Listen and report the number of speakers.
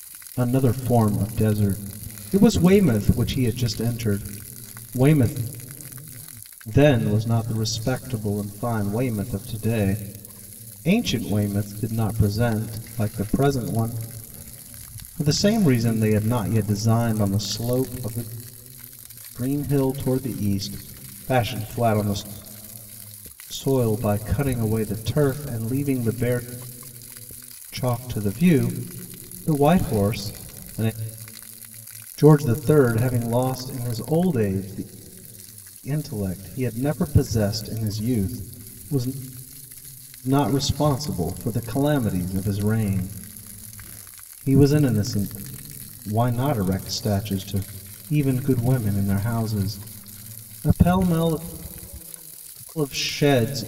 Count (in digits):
1